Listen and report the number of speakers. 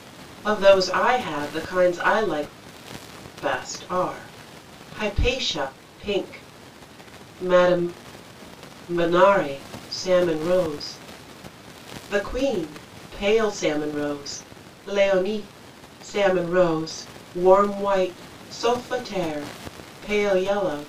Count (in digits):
1